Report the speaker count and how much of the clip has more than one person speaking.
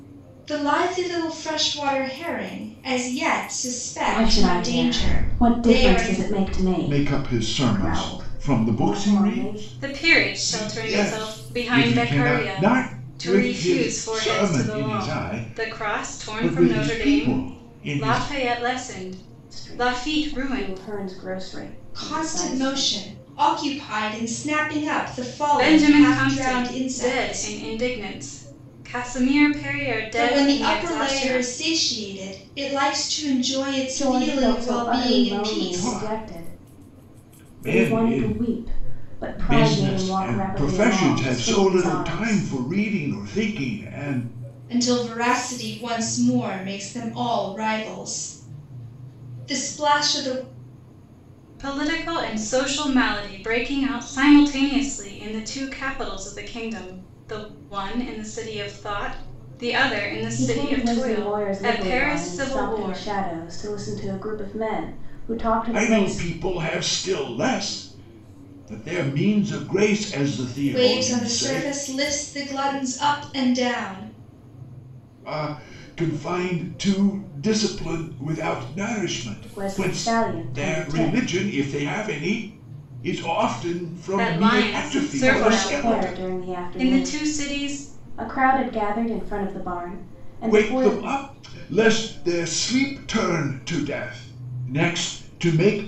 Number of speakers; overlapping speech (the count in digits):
4, about 38%